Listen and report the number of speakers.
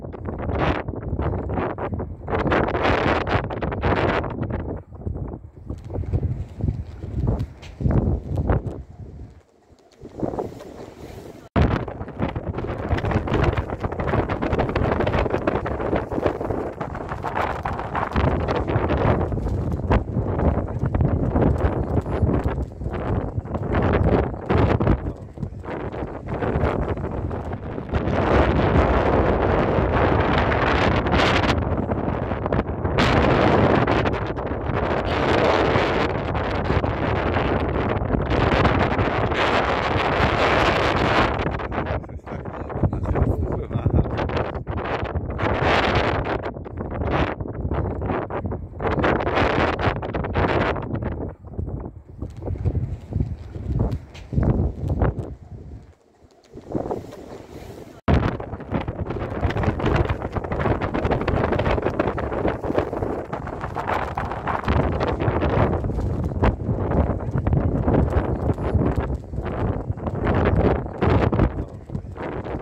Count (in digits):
0